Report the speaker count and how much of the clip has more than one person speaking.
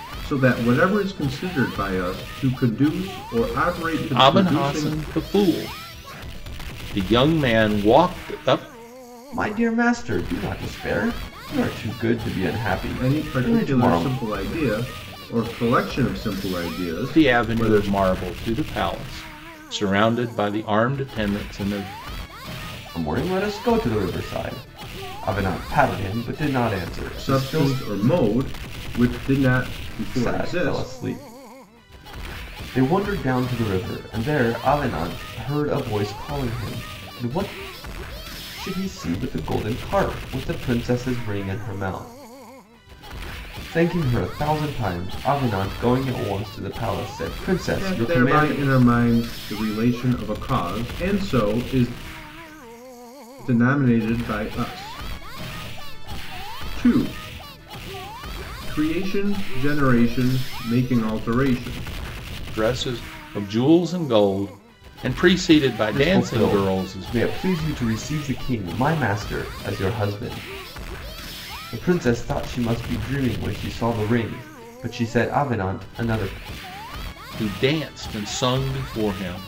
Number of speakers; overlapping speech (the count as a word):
three, about 8%